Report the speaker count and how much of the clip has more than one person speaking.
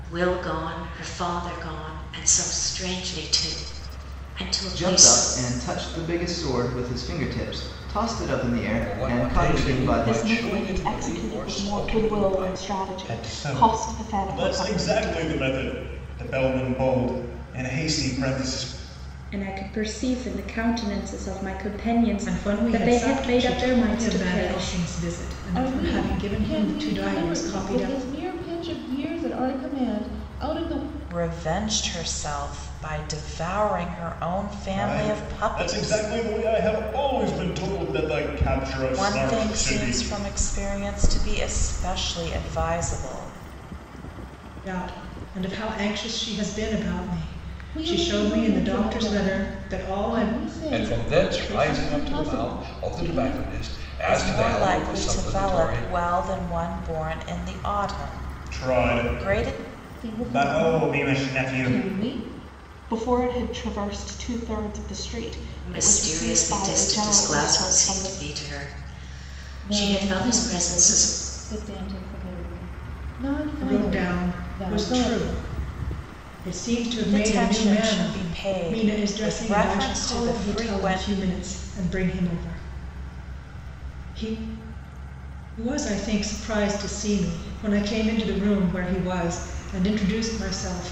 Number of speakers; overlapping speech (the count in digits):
9, about 37%